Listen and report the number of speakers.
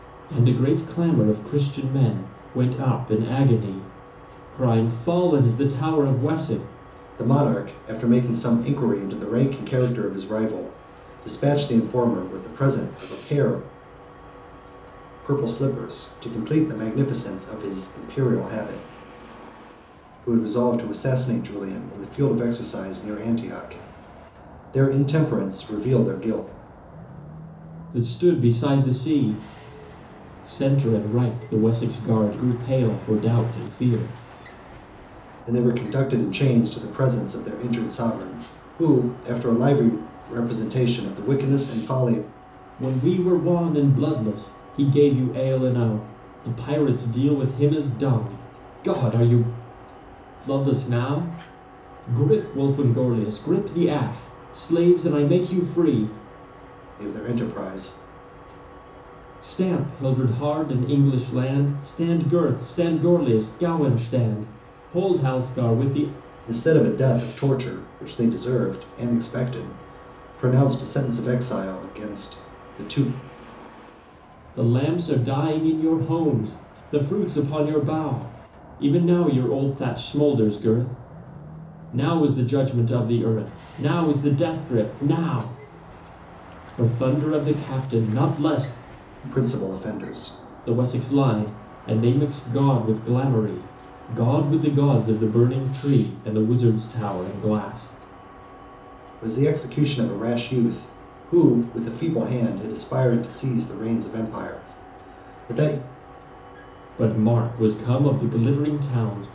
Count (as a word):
two